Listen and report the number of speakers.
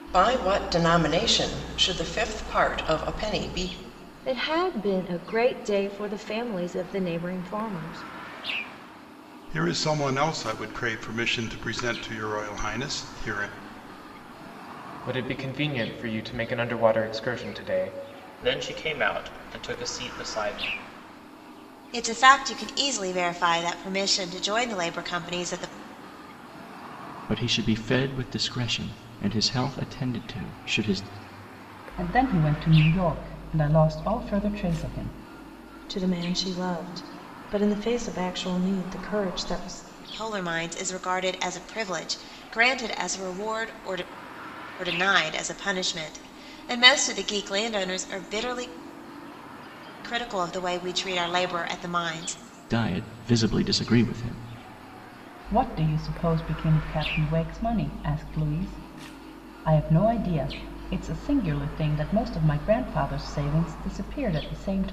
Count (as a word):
nine